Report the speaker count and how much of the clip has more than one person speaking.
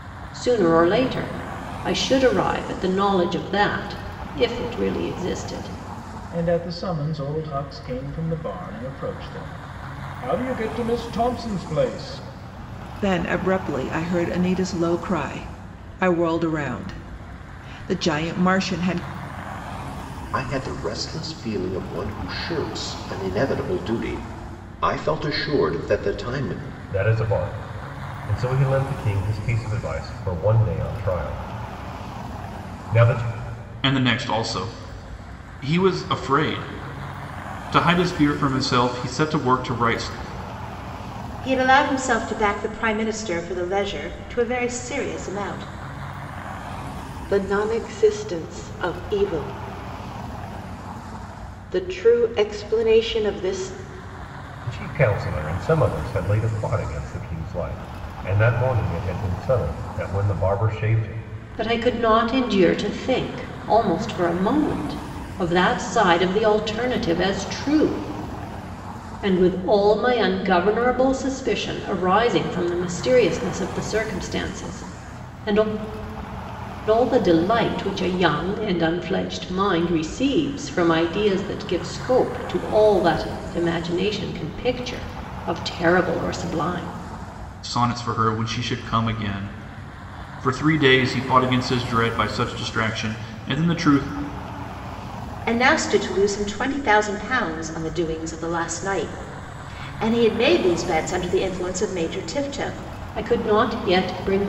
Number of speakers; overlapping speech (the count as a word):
eight, no overlap